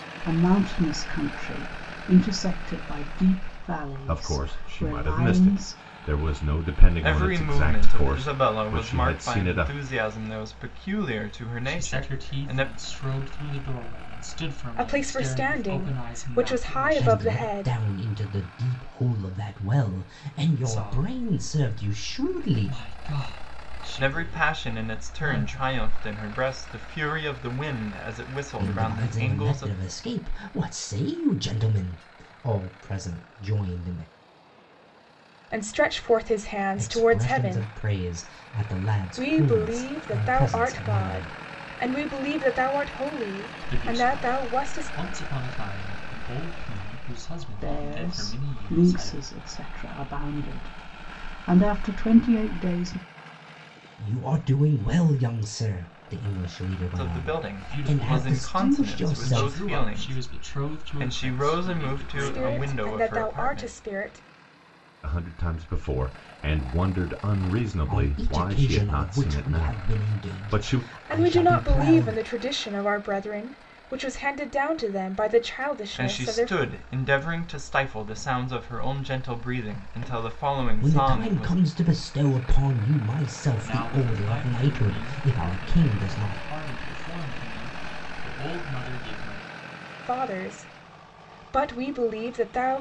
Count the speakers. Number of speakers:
6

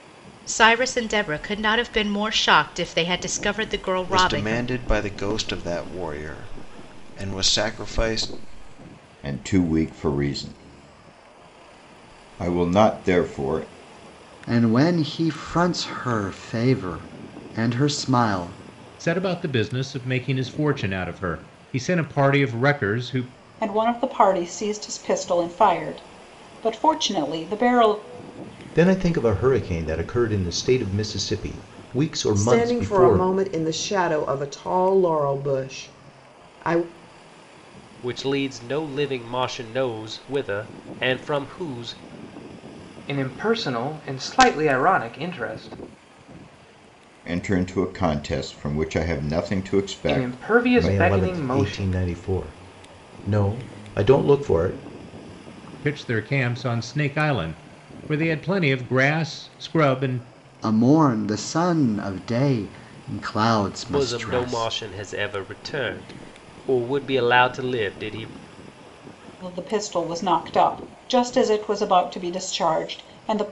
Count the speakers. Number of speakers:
10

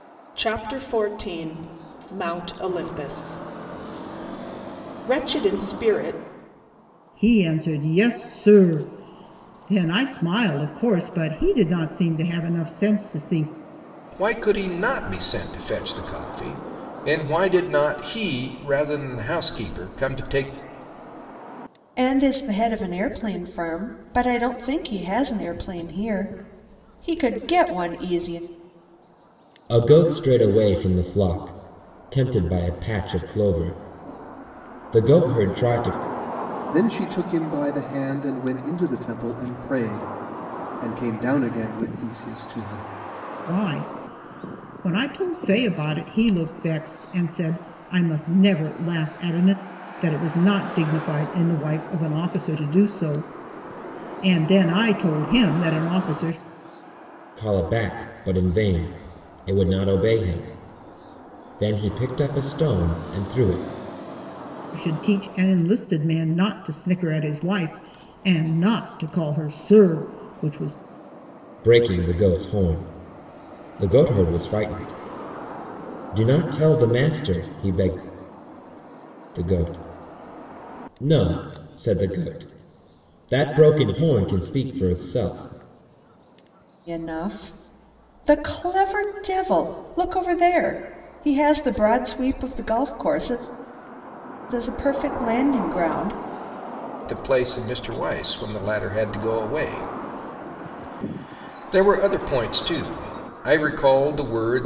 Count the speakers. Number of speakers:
6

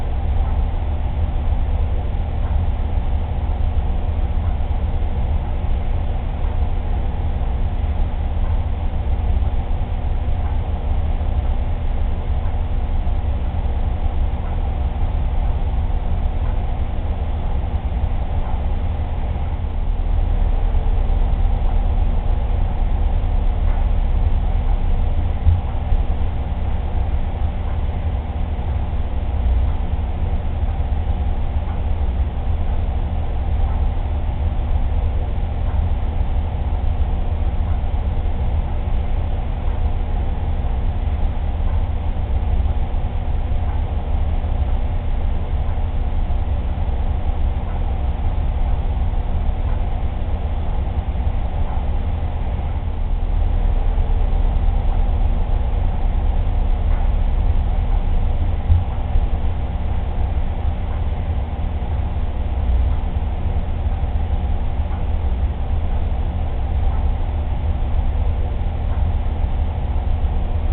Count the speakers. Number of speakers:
0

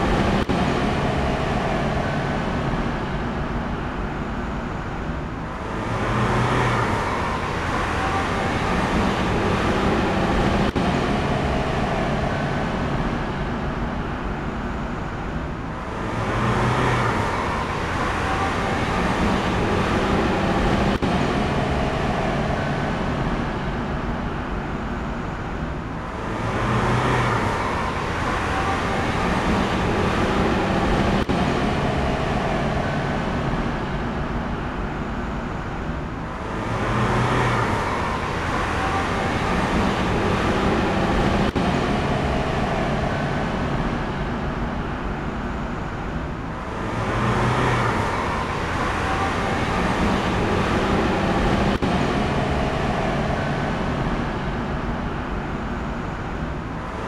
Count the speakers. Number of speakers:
0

